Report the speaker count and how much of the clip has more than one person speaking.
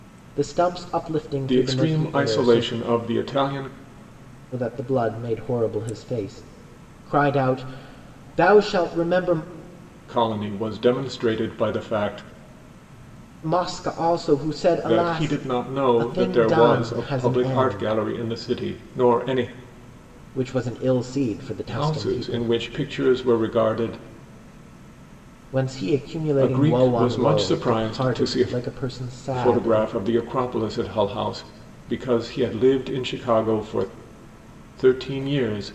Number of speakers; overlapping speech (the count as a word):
two, about 21%